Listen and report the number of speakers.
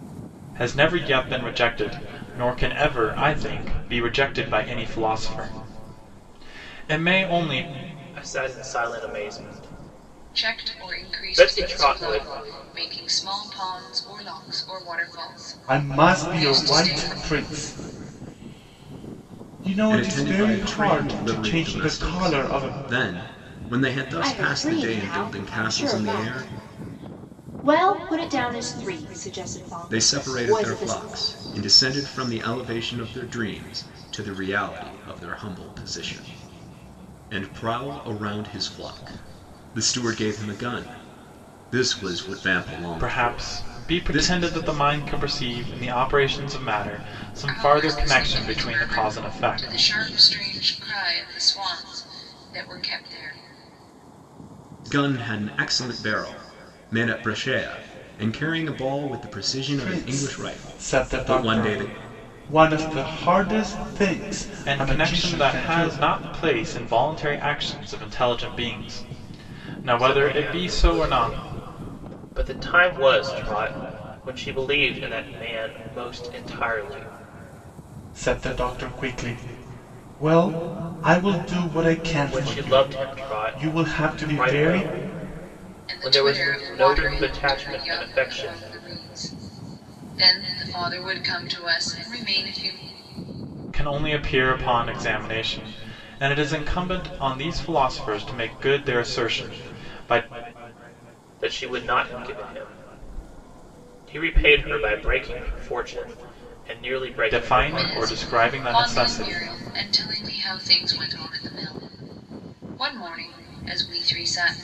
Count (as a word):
six